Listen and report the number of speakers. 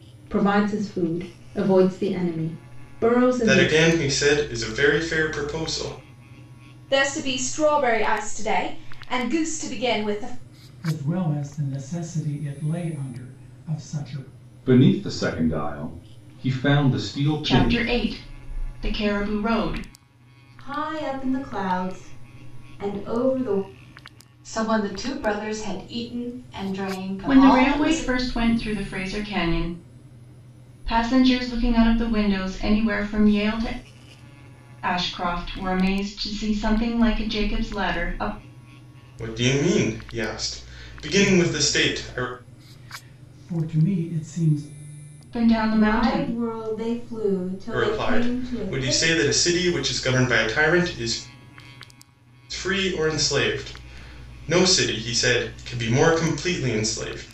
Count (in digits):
8